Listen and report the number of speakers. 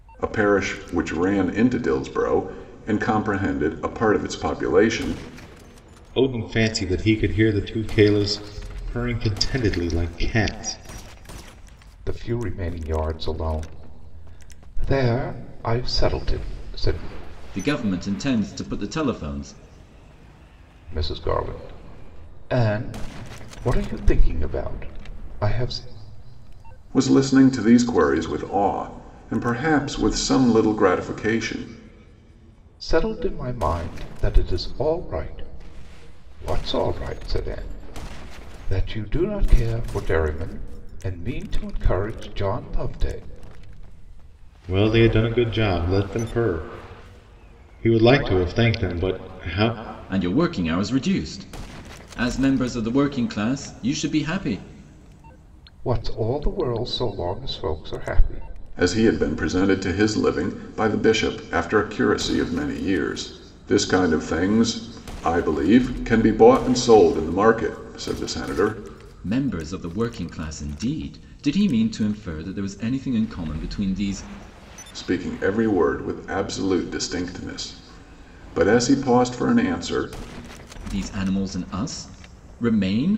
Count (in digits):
4